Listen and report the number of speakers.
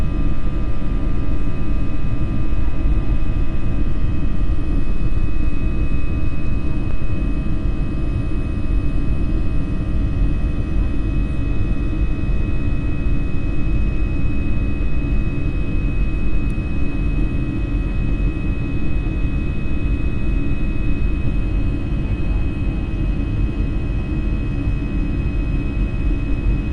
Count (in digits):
0